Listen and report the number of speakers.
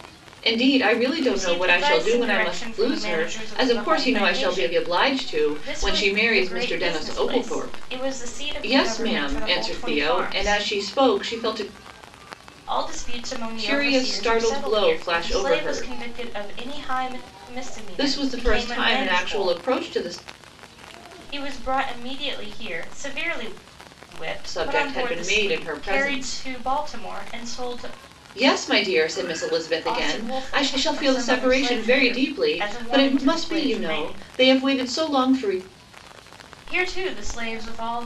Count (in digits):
2